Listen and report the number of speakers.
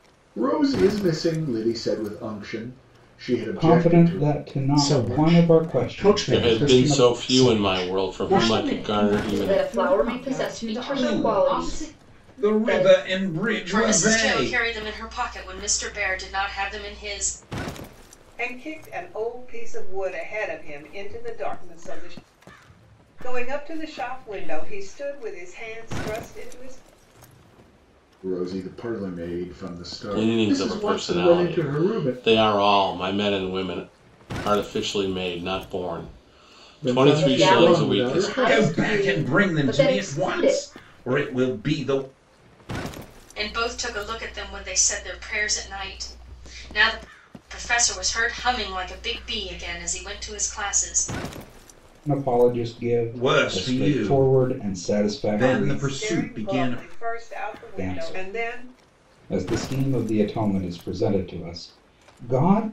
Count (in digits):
9